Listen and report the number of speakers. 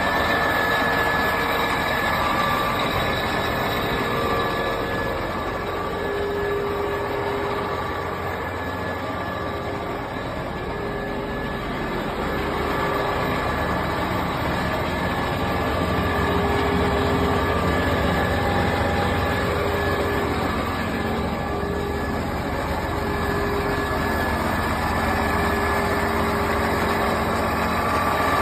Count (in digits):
0